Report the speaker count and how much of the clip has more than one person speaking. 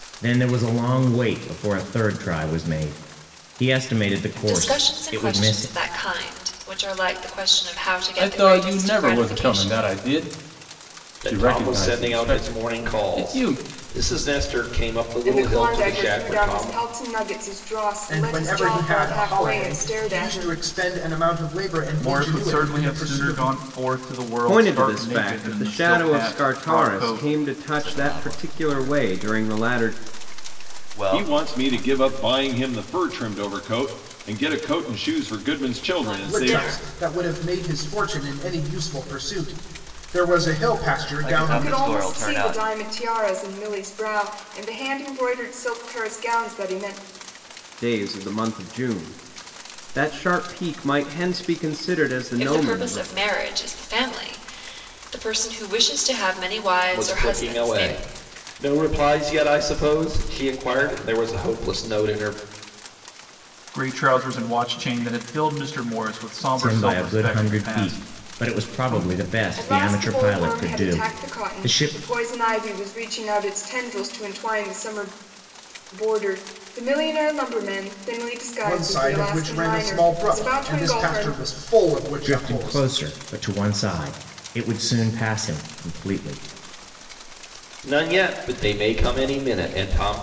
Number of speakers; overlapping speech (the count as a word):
ten, about 33%